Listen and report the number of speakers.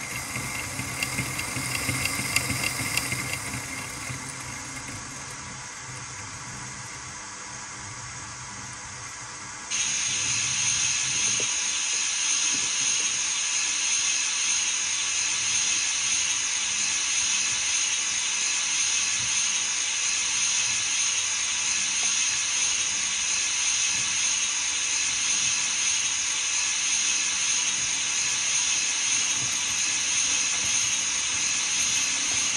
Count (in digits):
0